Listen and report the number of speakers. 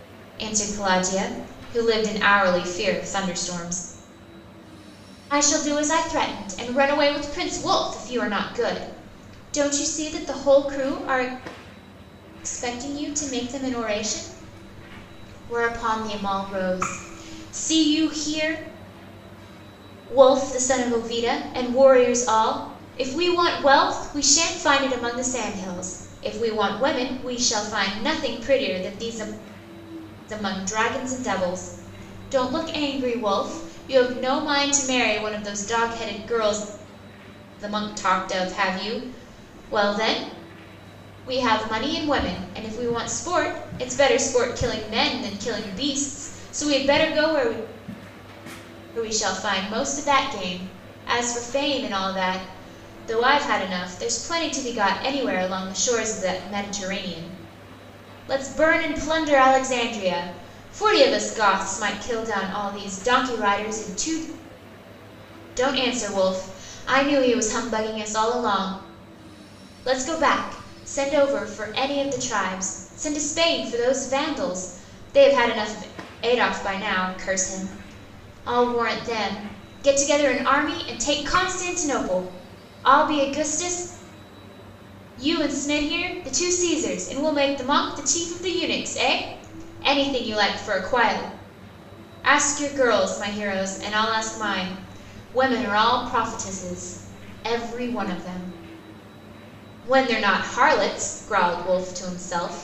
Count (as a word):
one